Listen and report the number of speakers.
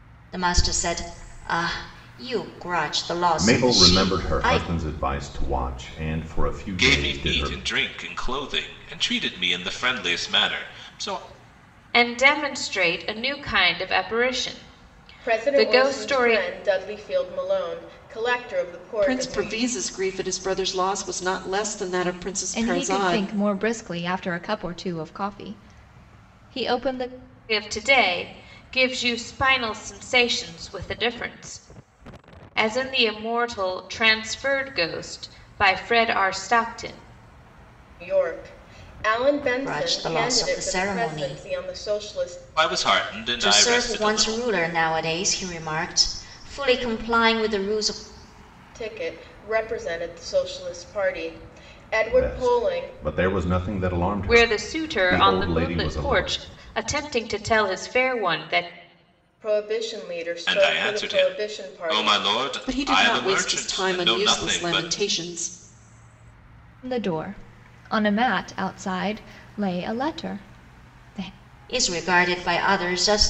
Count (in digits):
7